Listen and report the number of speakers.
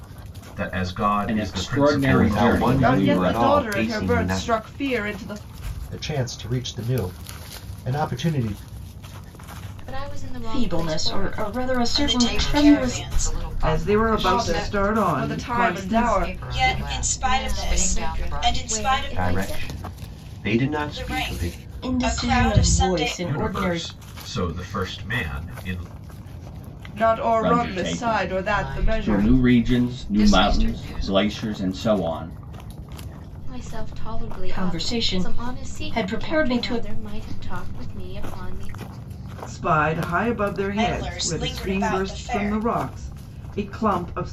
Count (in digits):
10